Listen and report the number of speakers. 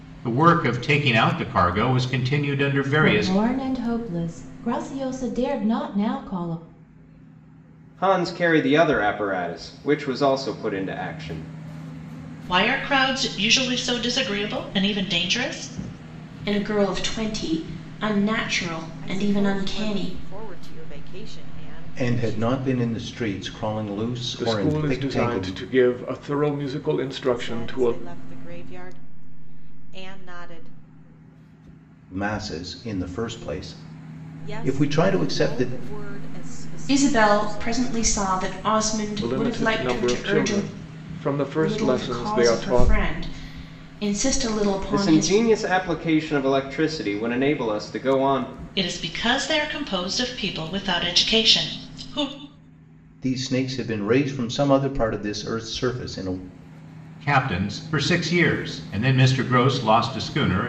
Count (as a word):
eight